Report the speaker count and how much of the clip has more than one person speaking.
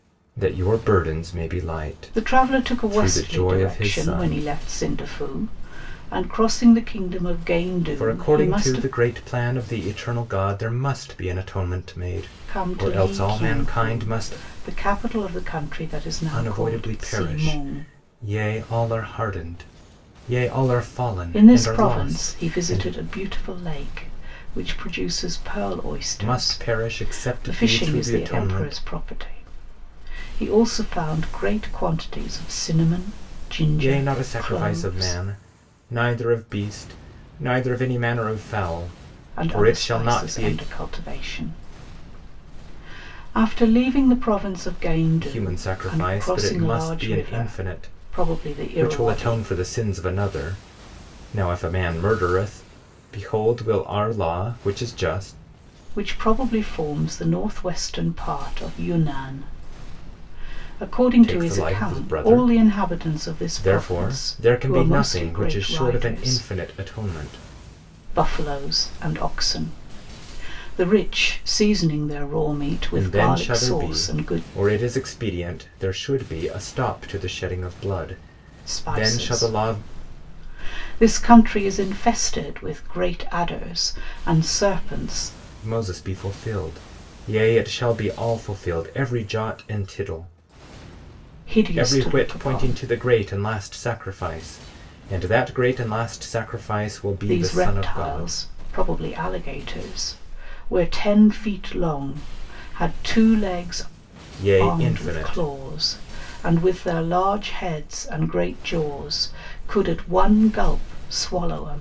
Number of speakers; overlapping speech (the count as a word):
two, about 25%